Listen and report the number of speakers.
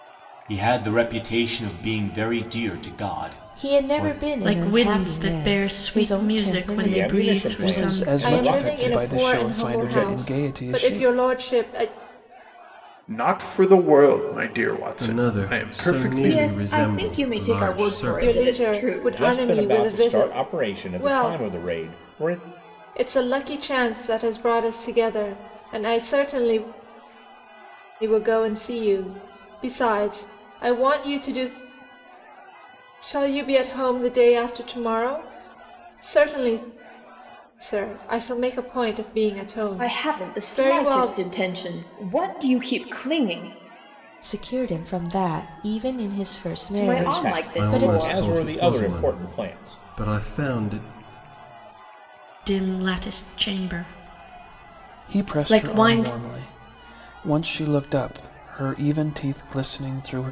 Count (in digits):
9